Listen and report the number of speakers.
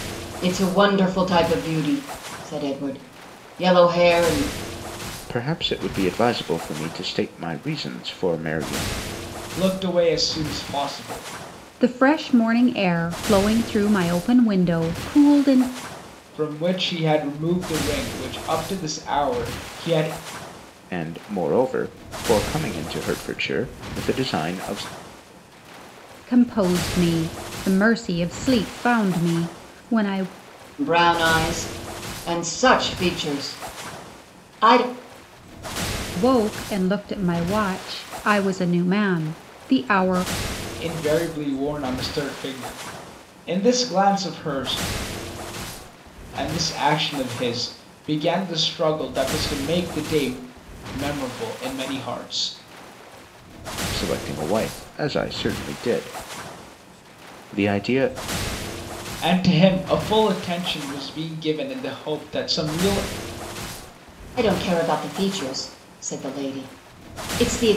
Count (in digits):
4